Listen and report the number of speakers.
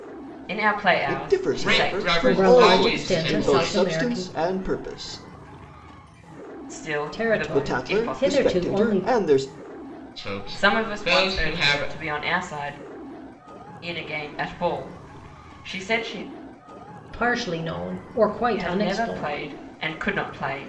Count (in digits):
4